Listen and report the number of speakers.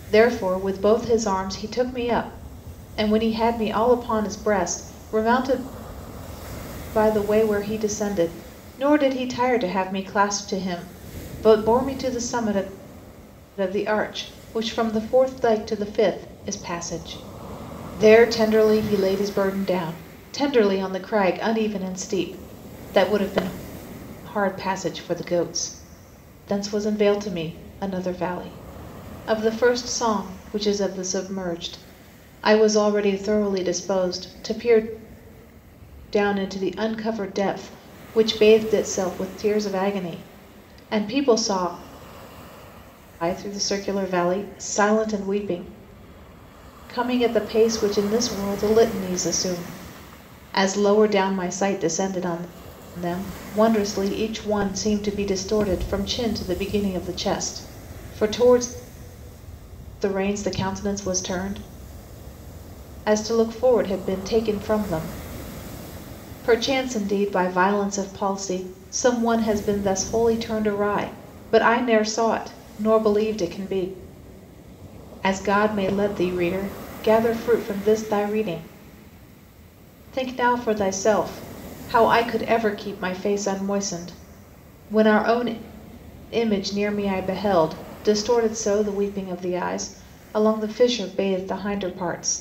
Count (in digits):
1